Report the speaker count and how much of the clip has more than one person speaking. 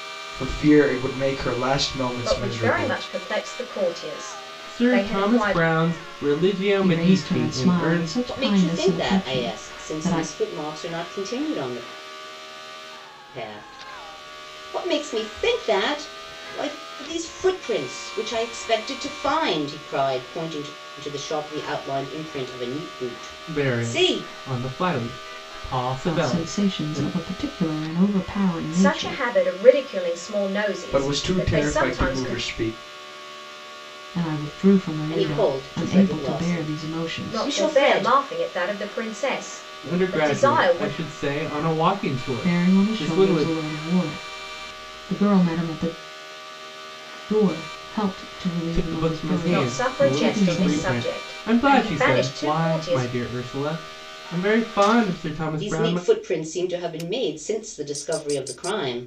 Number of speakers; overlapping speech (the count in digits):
5, about 34%